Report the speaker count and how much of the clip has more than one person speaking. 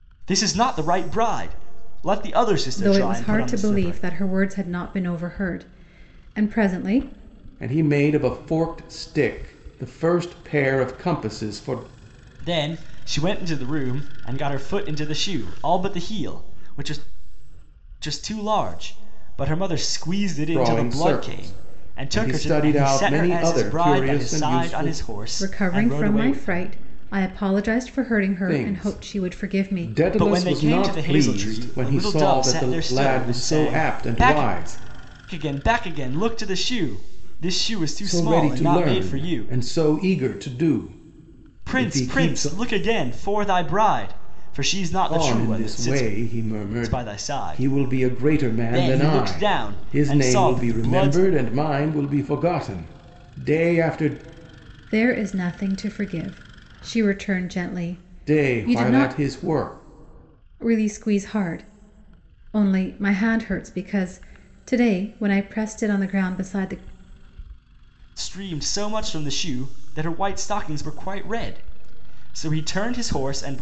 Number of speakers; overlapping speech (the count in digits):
3, about 29%